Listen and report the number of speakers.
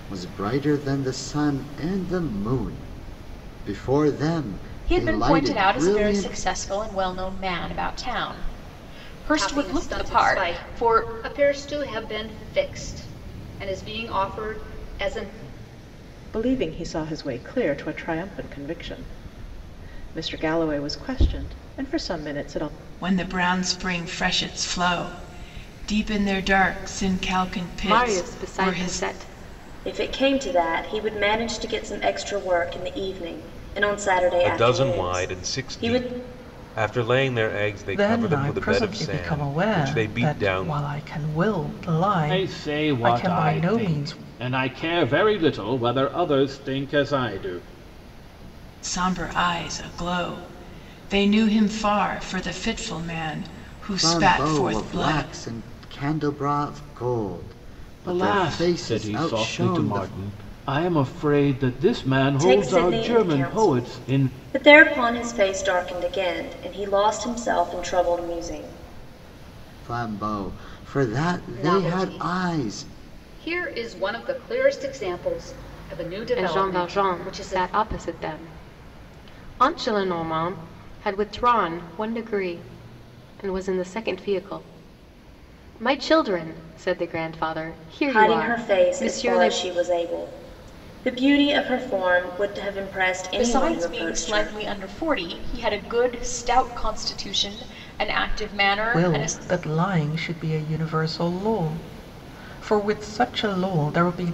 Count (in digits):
10